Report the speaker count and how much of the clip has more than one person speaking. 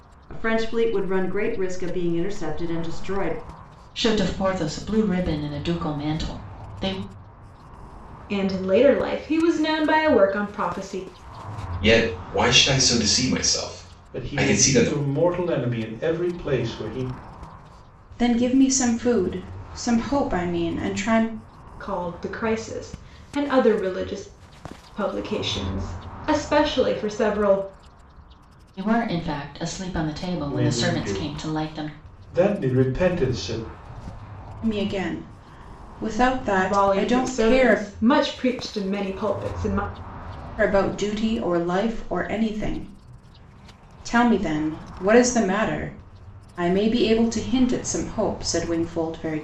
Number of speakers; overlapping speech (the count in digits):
6, about 7%